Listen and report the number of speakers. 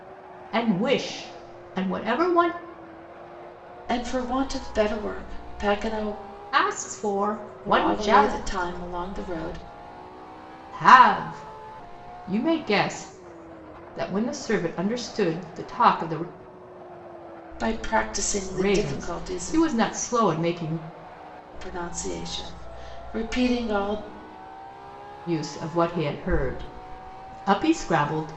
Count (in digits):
2